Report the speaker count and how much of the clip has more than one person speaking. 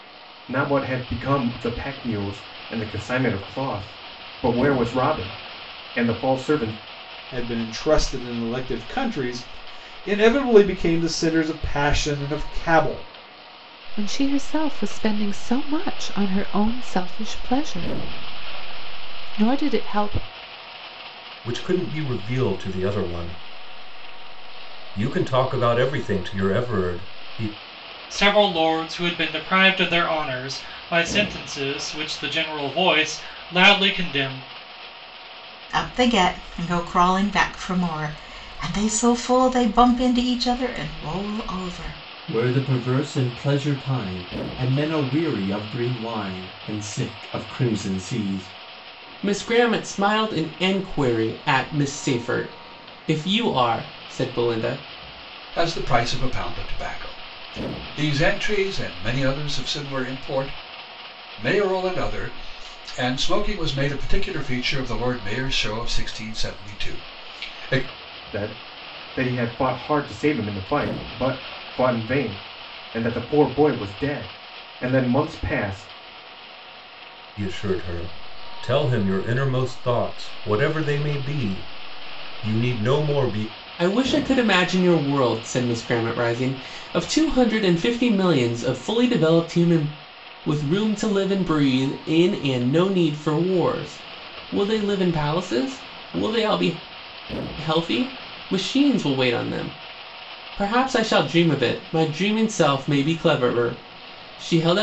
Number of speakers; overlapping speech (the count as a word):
nine, no overlap